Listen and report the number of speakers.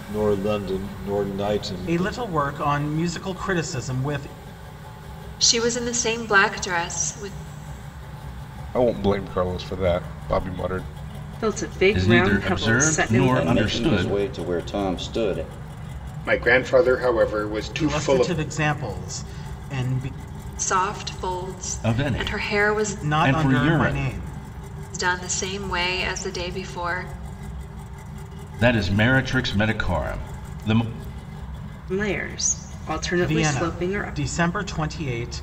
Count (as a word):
eight